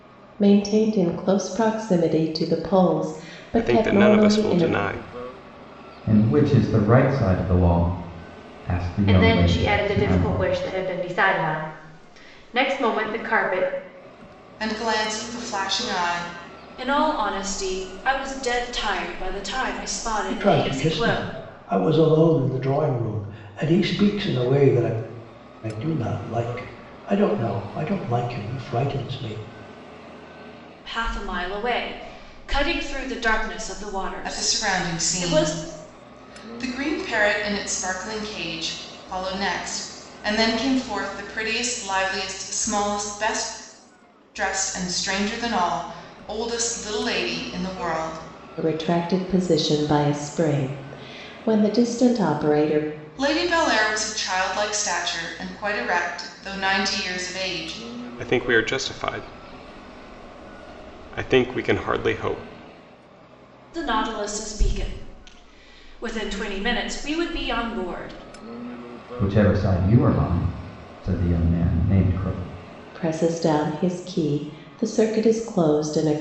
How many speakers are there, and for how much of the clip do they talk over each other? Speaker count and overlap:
seven, about 7%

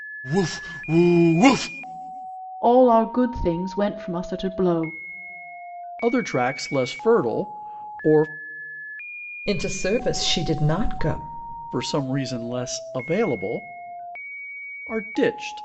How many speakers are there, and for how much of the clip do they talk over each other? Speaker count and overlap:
four, no overlap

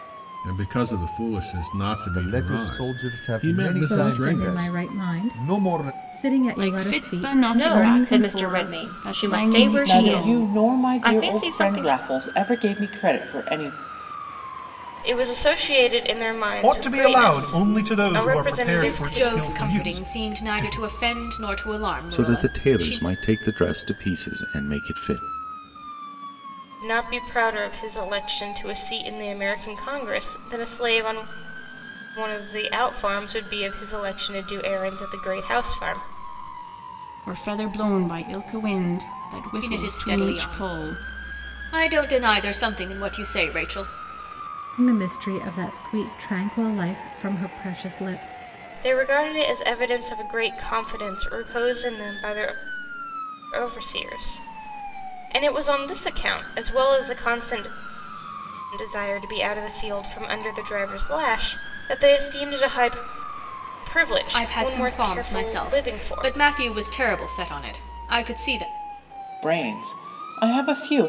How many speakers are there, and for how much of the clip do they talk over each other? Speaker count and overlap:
ten, about 25%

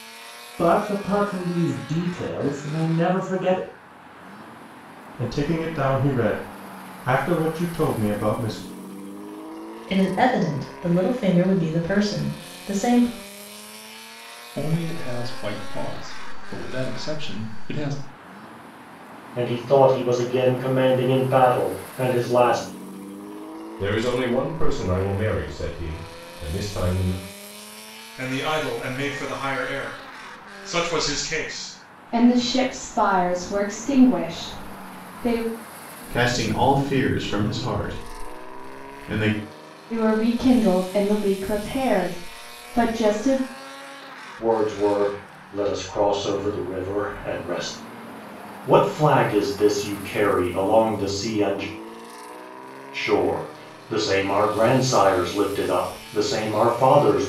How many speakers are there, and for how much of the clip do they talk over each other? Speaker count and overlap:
nine, no overlap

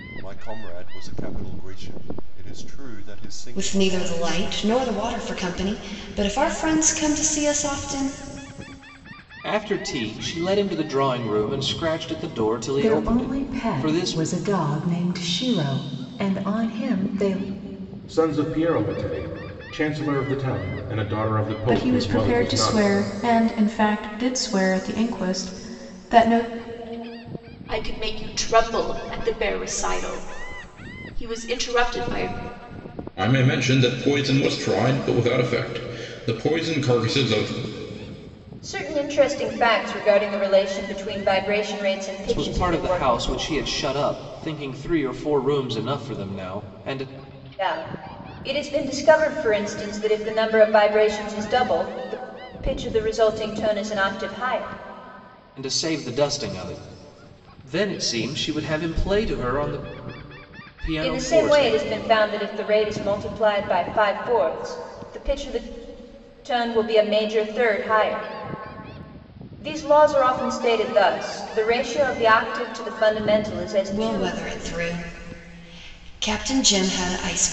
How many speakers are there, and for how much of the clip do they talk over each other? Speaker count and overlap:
nine, about 8%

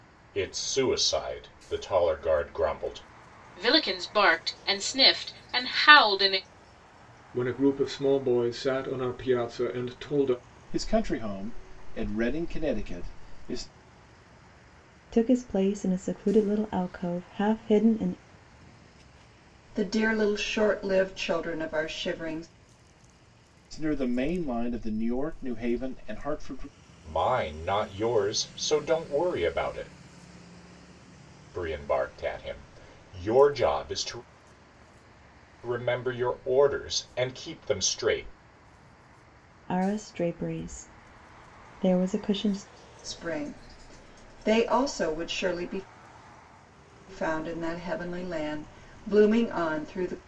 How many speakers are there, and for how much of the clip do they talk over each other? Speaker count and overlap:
six, no overlap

